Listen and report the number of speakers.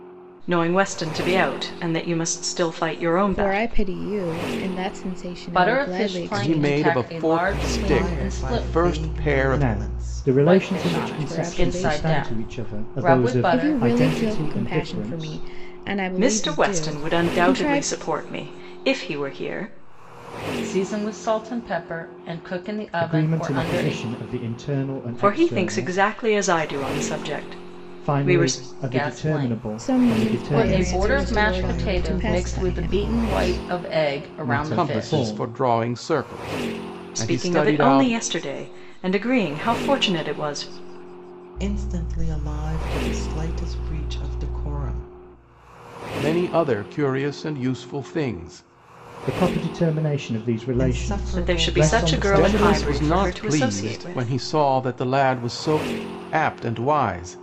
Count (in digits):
6